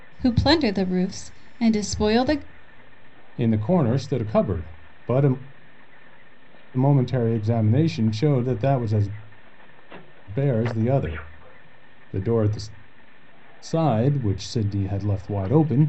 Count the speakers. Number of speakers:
2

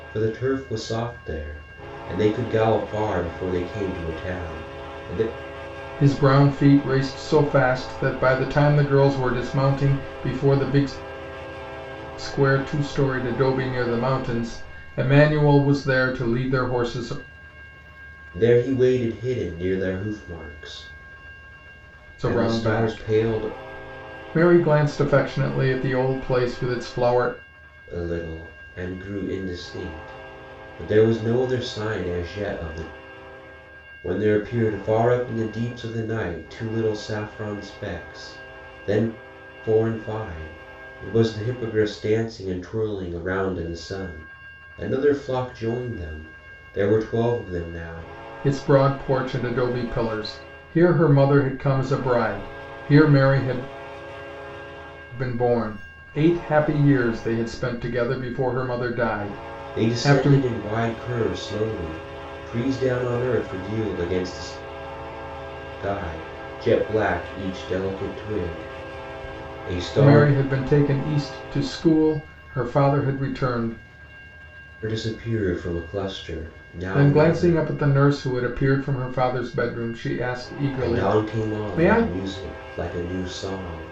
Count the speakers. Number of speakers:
2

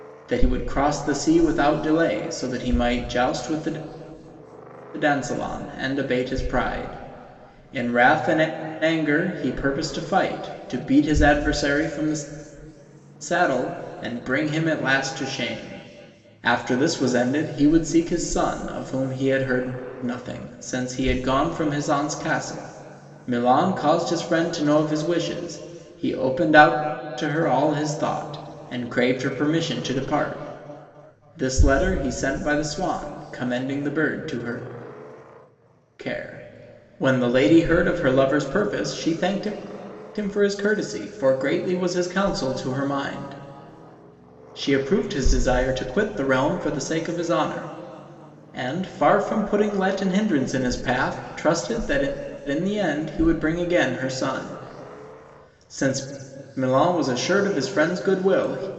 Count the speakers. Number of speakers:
1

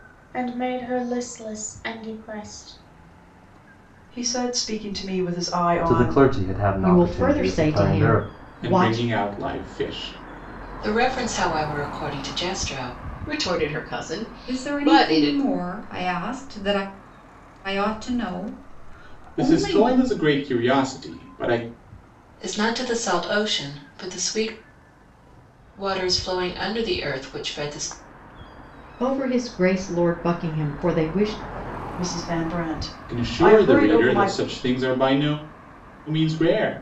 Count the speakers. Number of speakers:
8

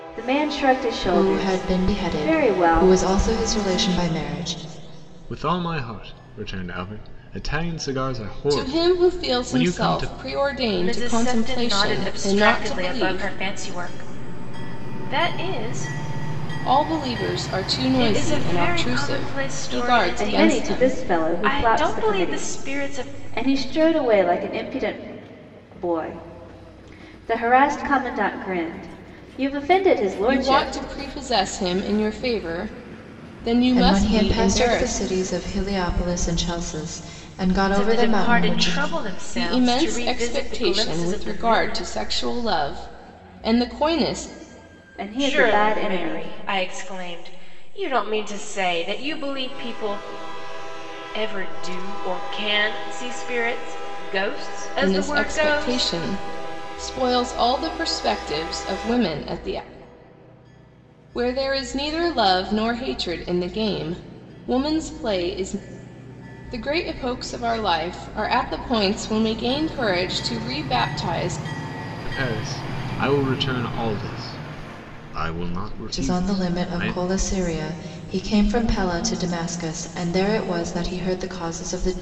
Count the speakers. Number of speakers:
5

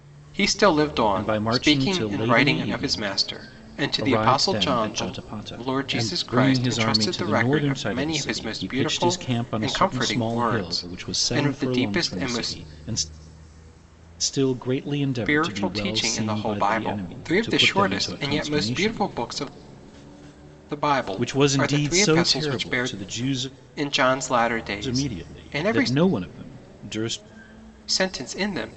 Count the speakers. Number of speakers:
2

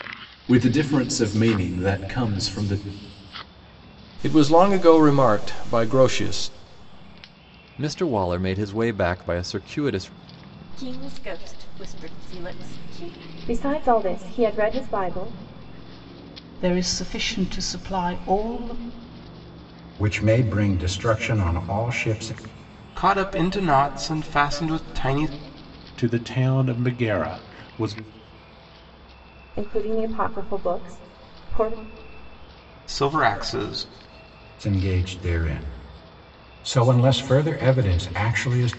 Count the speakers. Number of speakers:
9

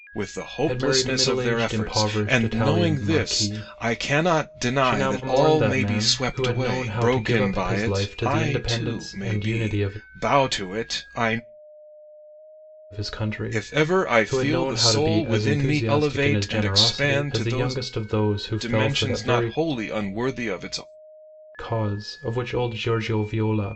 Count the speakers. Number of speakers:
2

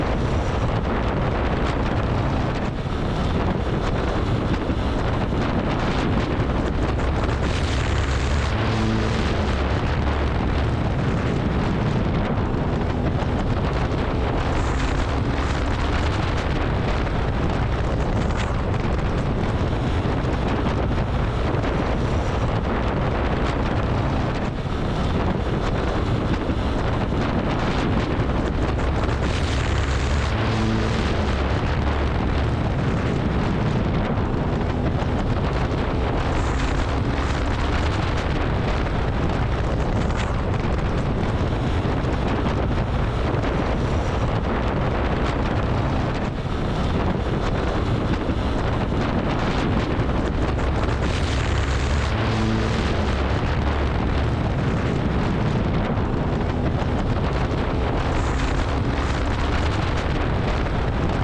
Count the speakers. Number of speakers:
0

